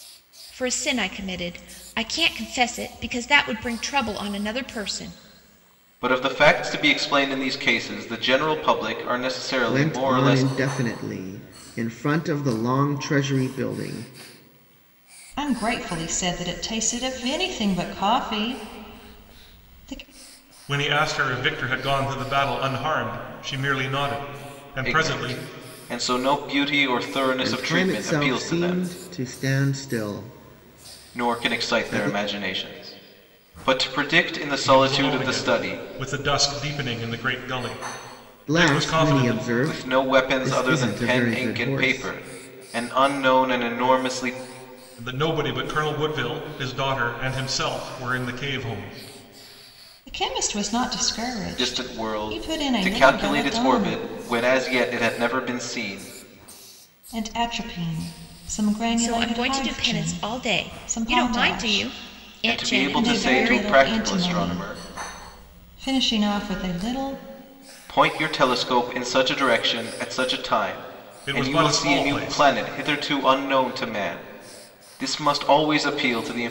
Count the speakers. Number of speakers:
5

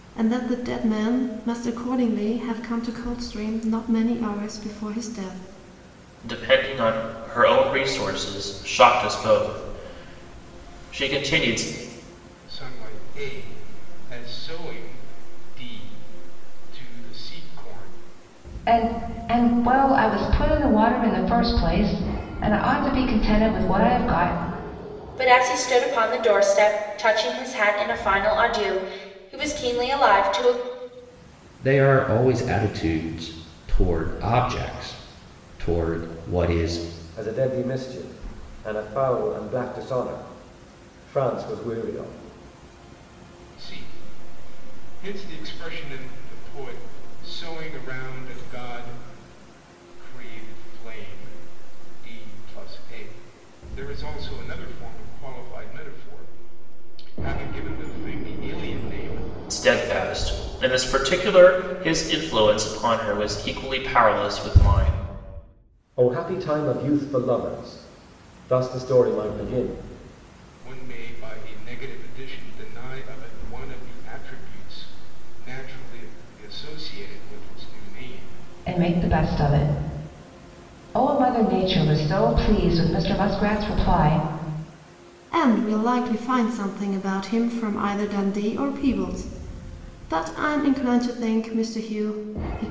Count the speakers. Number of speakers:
7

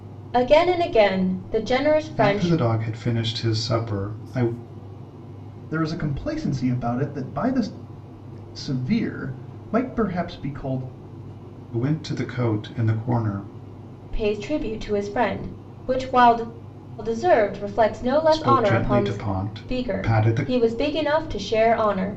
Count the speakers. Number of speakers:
3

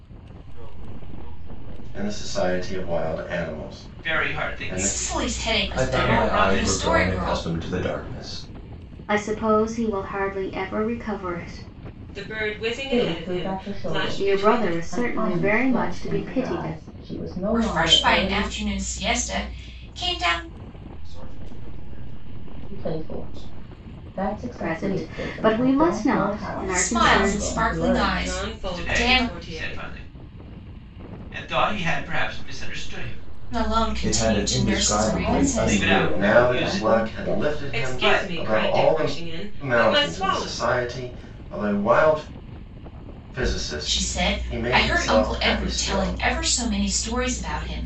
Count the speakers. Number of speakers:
8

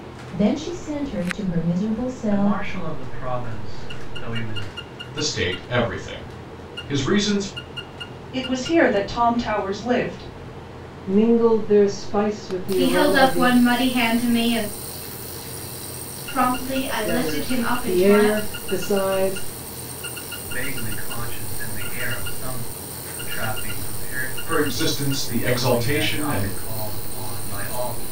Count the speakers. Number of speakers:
6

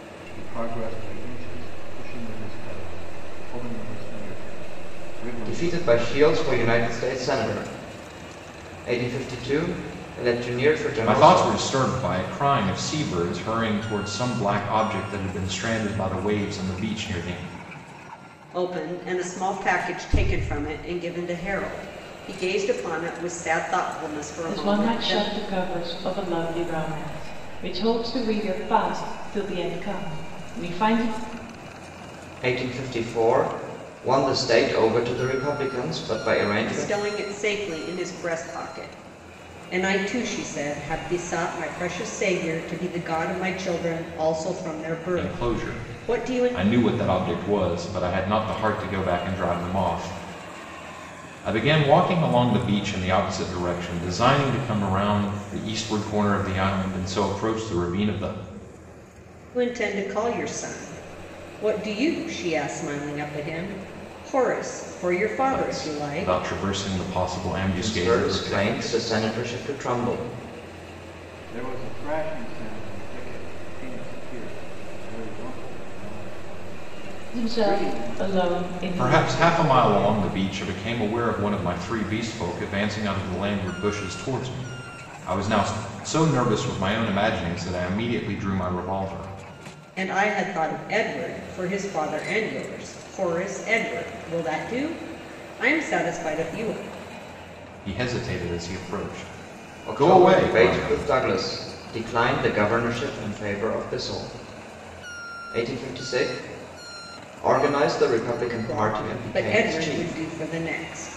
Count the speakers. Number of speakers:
5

